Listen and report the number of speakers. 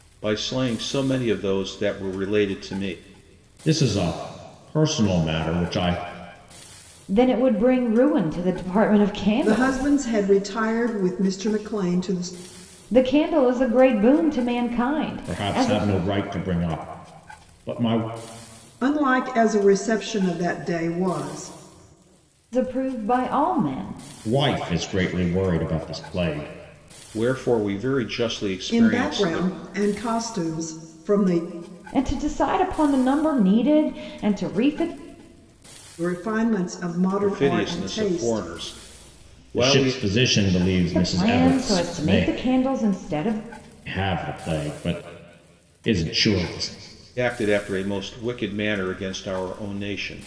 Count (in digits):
4